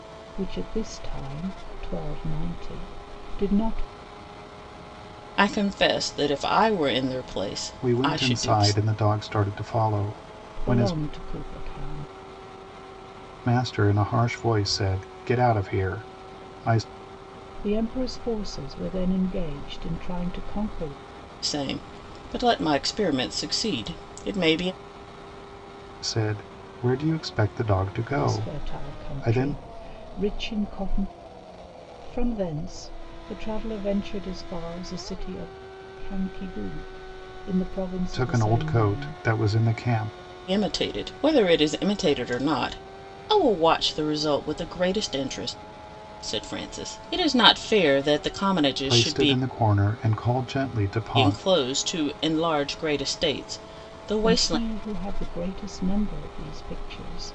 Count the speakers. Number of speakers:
3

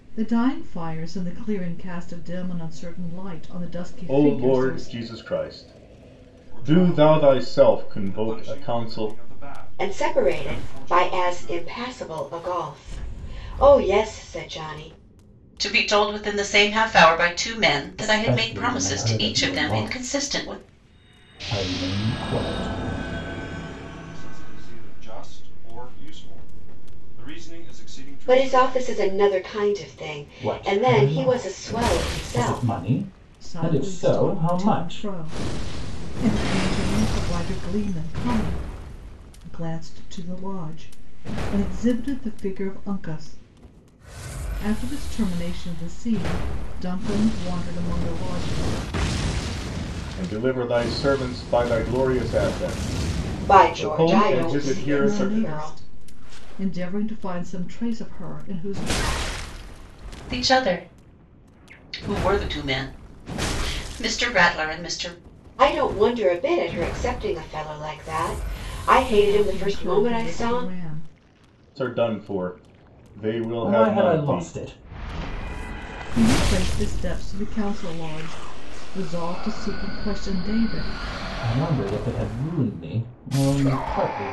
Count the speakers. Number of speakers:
6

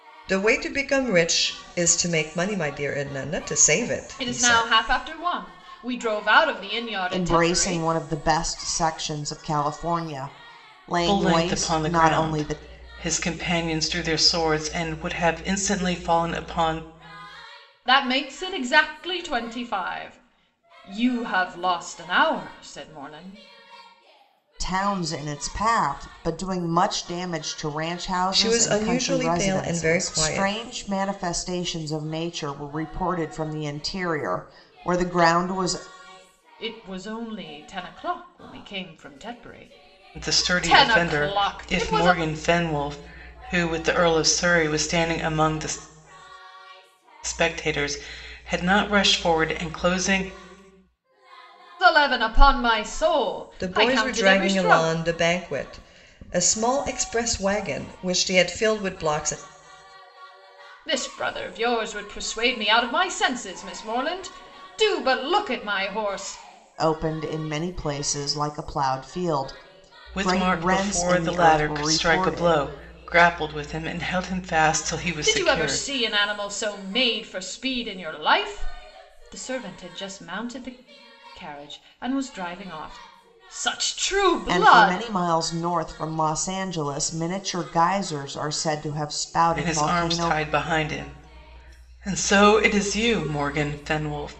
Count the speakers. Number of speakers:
4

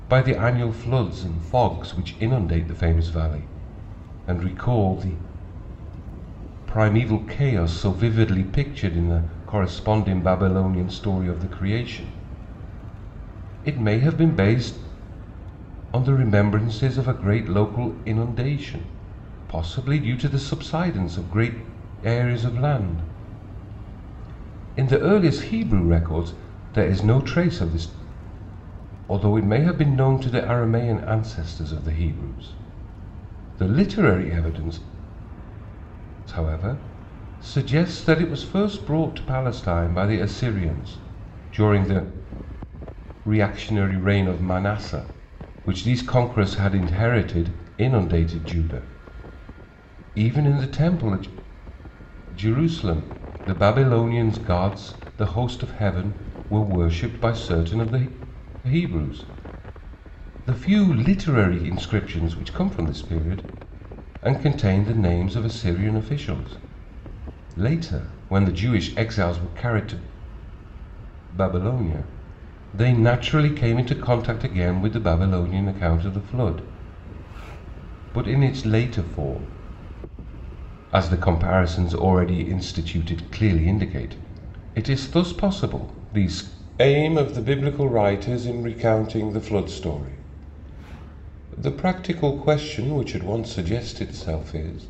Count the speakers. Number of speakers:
1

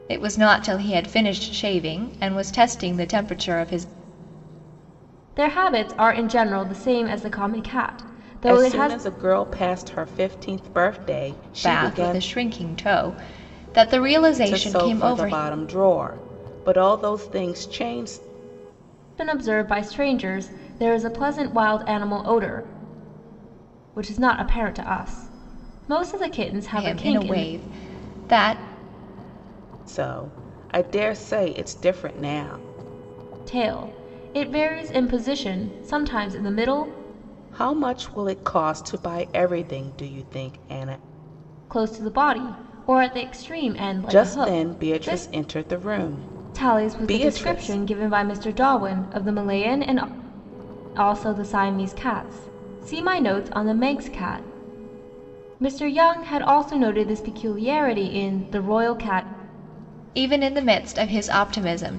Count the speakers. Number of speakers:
3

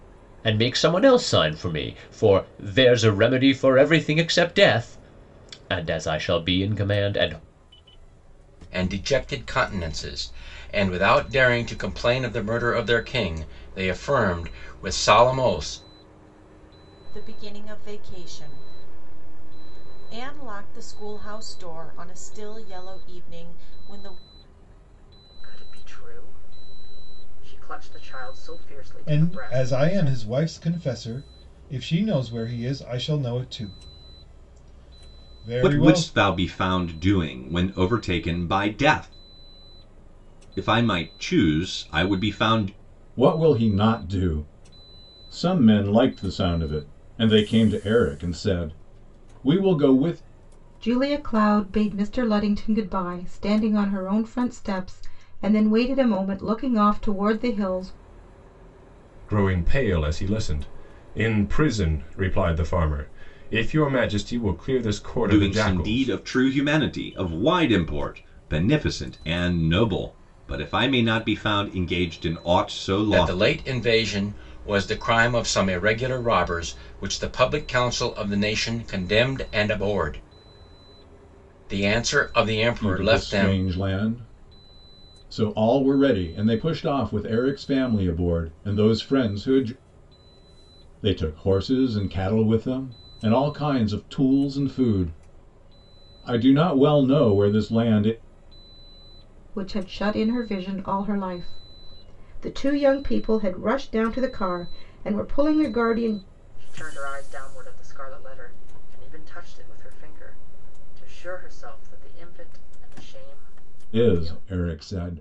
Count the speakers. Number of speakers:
9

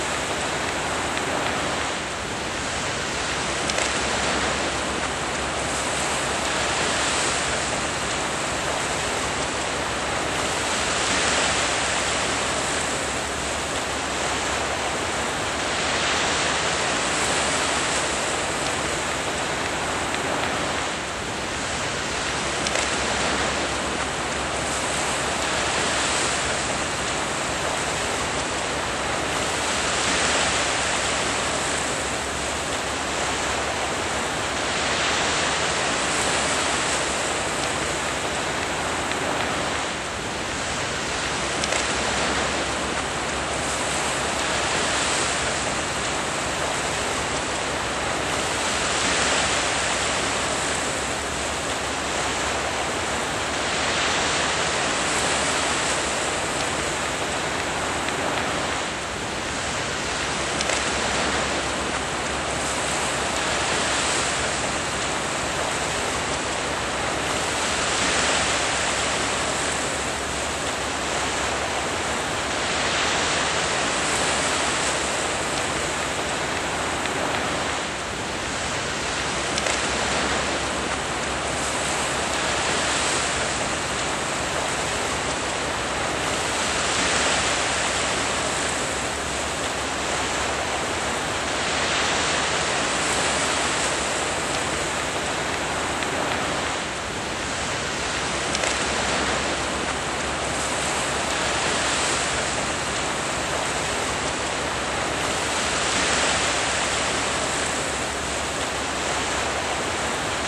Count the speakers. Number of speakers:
0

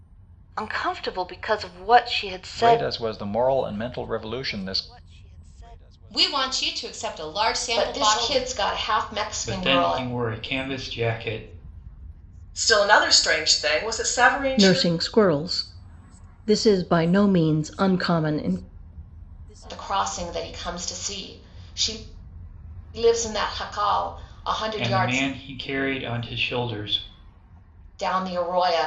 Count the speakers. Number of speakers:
7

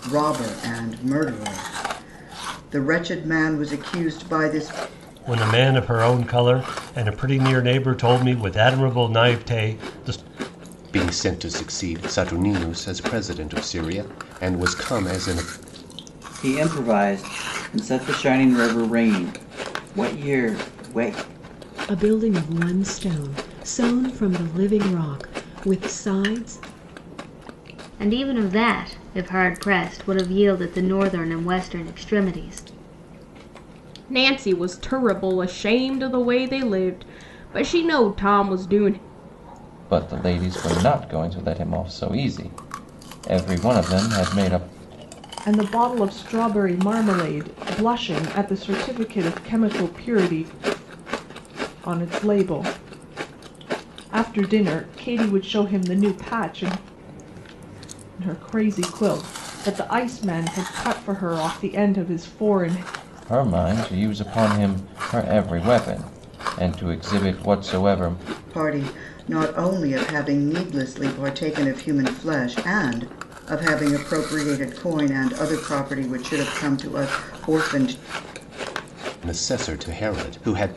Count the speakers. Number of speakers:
9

